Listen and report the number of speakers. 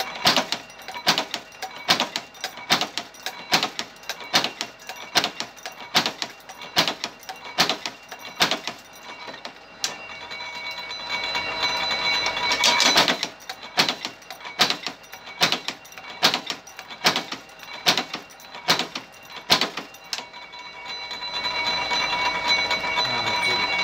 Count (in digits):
0